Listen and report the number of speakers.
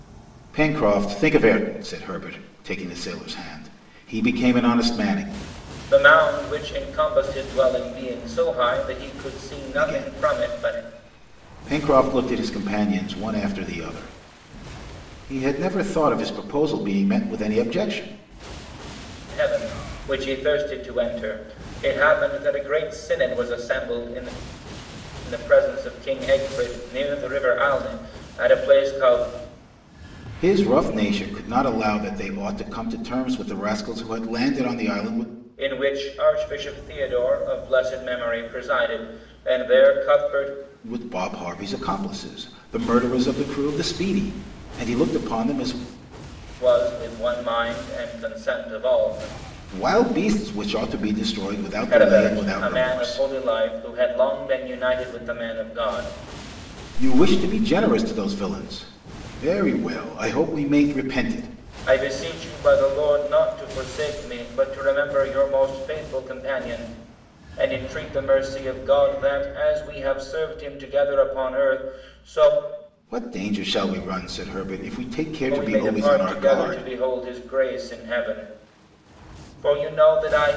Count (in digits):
2